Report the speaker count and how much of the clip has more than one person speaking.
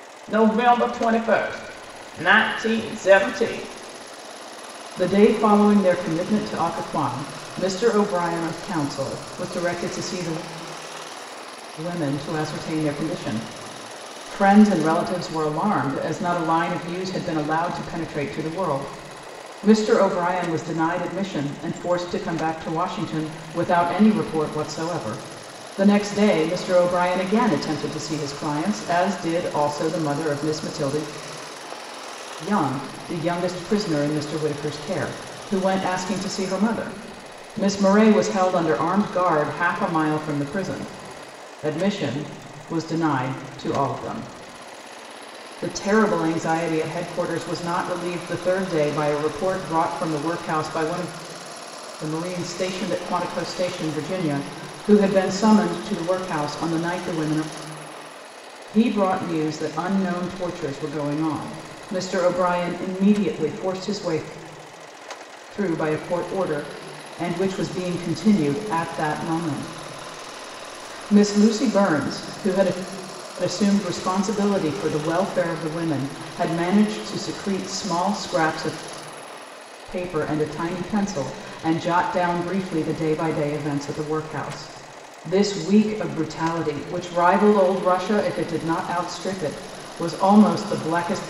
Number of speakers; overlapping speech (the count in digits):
1, no overlap